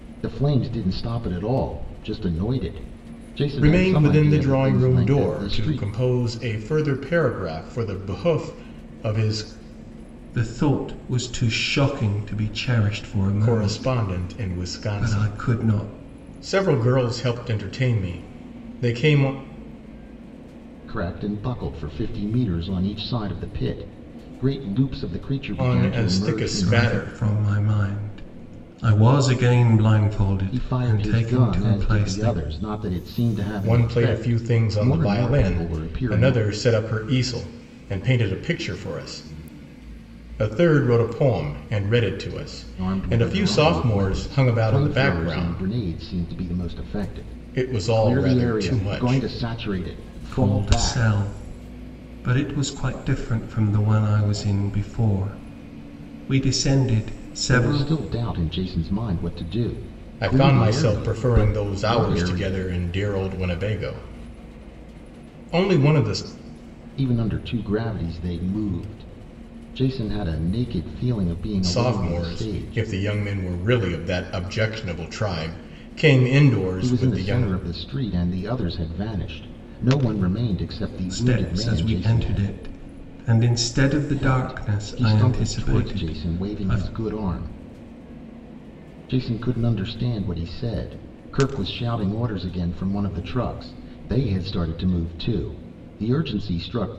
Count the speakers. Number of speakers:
3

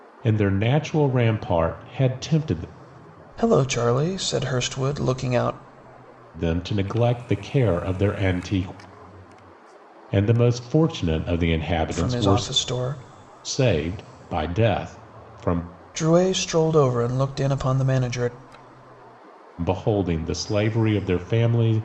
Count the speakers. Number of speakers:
2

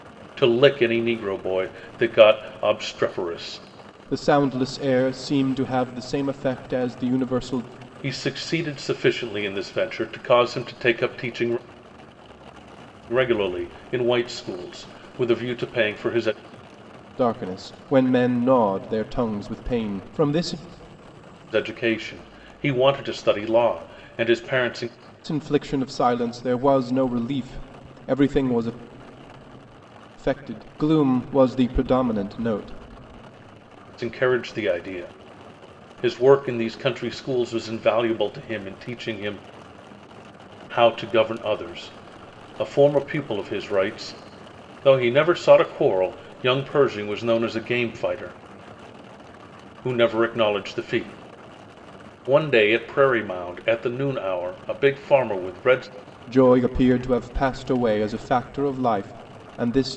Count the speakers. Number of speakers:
2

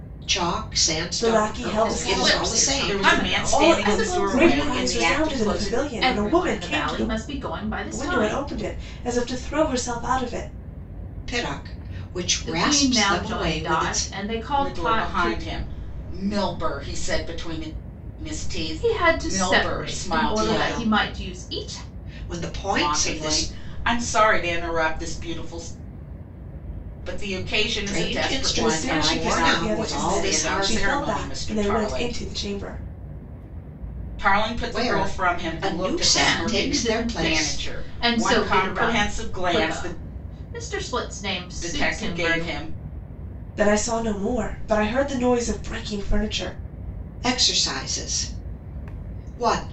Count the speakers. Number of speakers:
4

